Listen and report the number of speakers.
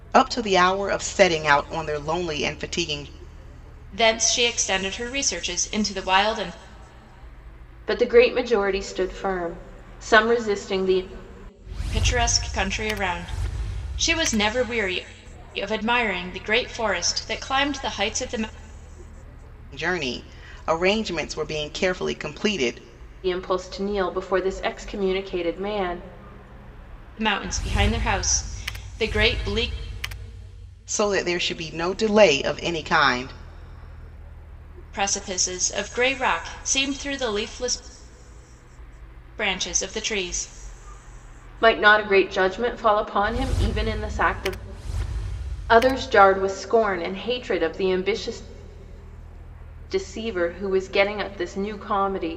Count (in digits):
3